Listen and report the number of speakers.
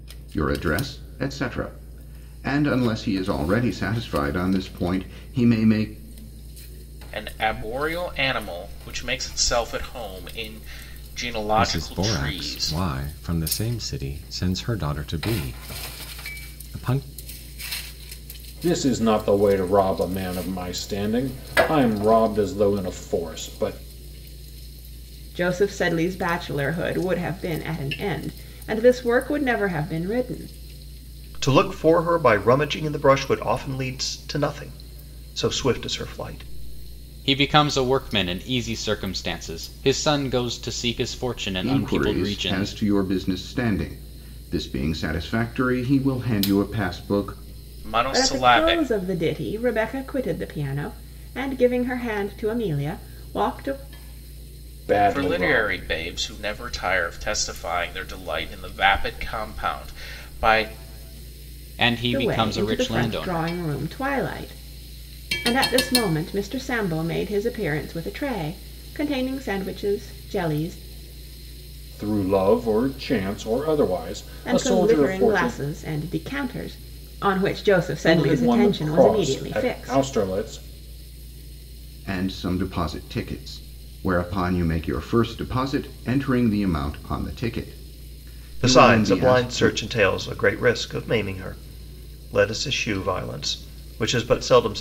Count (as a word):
seven